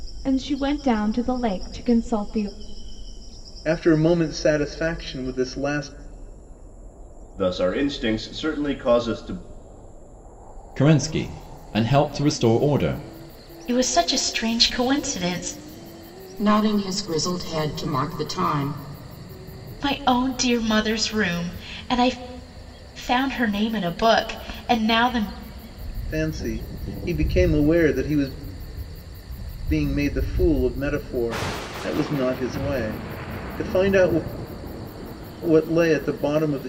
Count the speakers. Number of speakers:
6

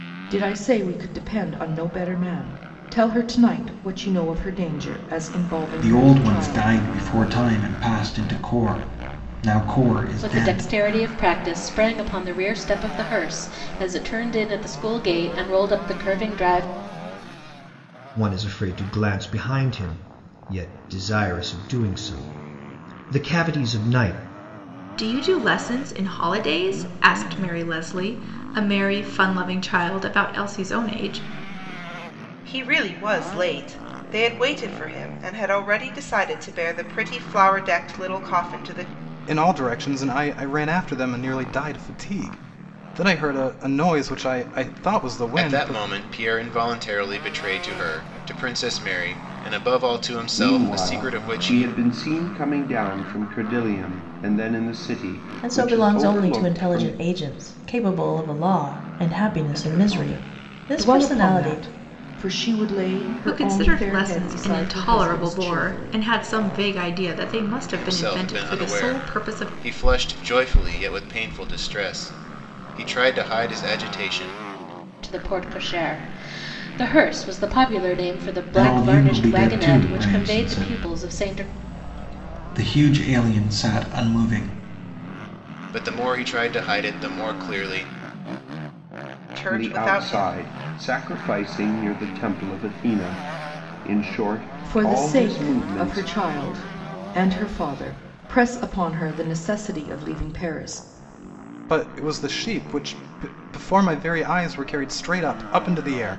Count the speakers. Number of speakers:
10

